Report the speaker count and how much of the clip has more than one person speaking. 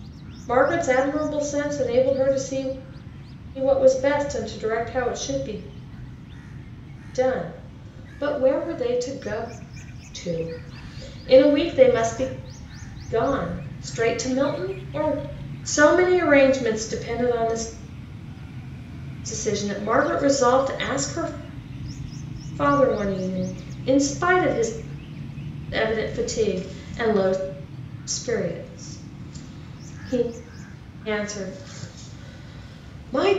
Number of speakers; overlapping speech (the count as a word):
one, no overlap